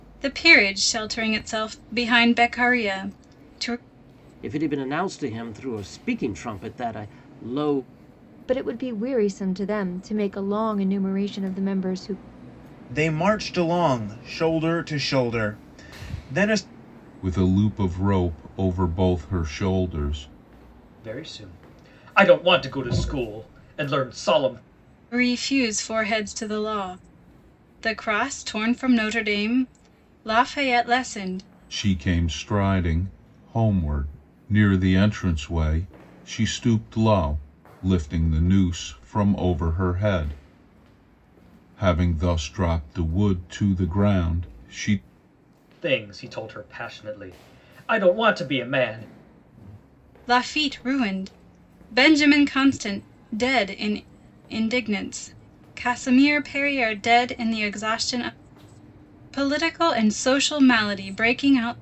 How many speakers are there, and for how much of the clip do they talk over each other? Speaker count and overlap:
6, no overlap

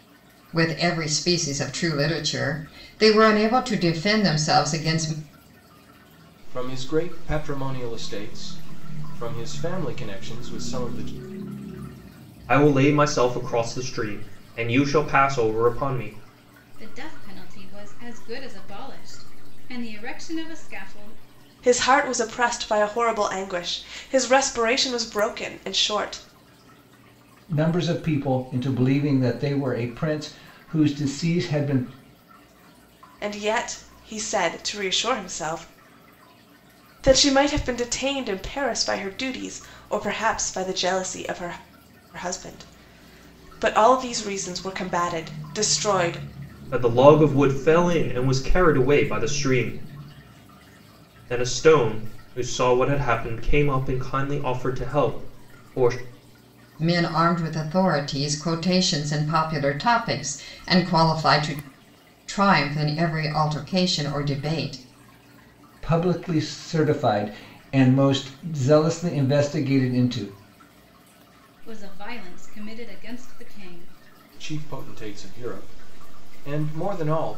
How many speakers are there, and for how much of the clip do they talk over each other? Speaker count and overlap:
6, no overlap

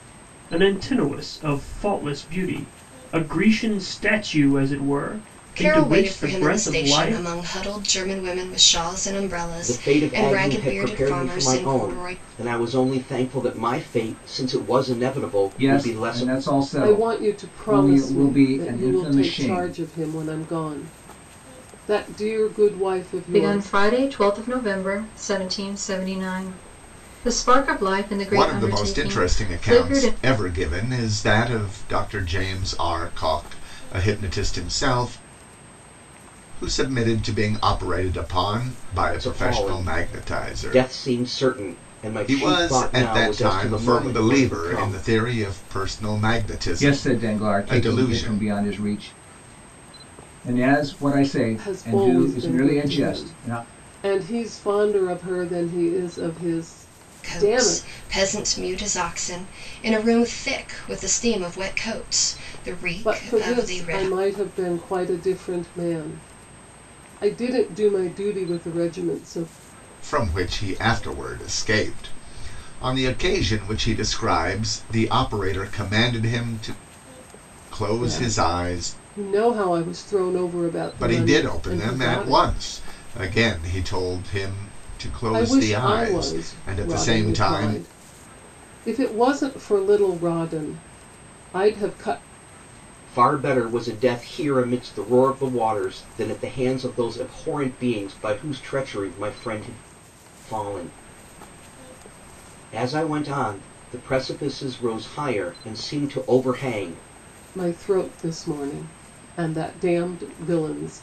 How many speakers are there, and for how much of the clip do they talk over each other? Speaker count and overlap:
7, about 23%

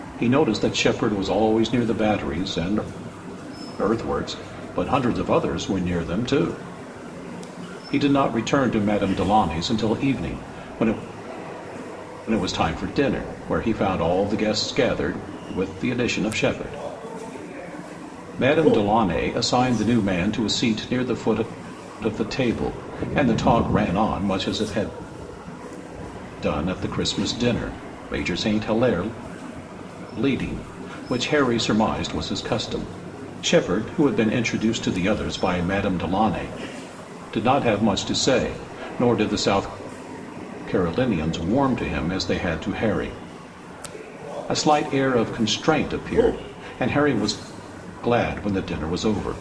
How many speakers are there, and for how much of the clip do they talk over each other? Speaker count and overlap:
1, no overlap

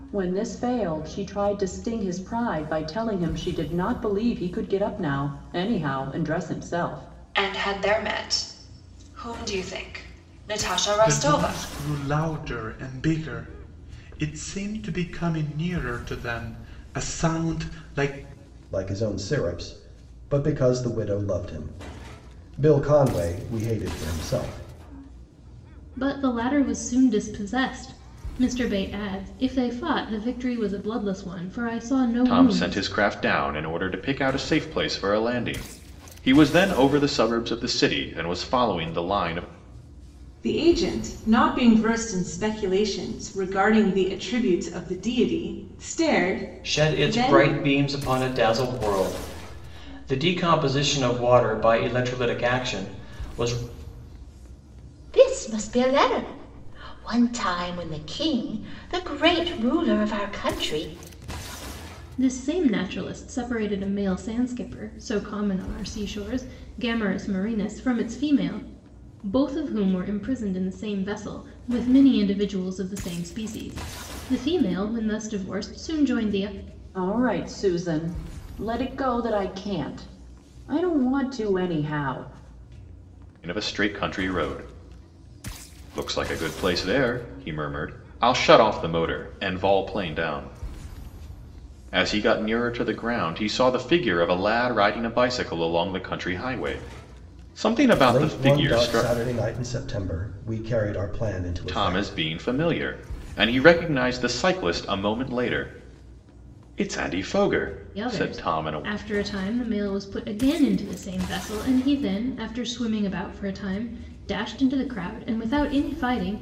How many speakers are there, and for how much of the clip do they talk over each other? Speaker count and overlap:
9, about 4%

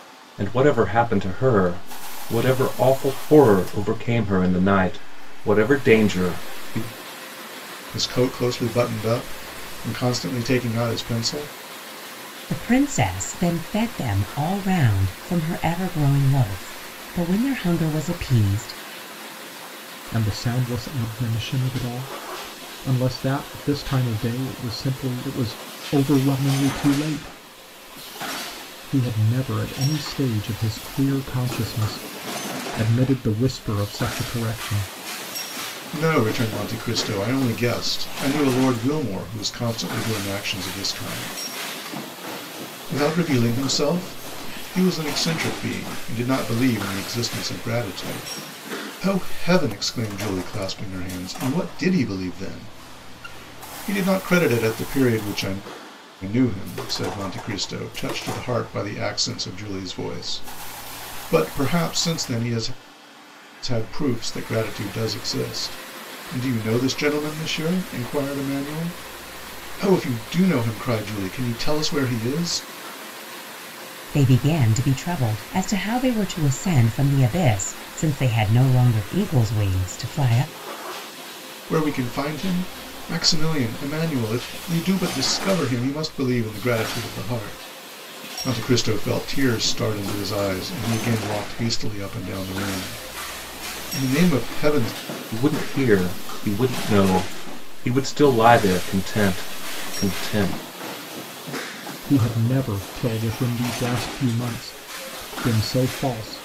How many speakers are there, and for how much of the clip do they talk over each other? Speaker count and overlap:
4, no overlap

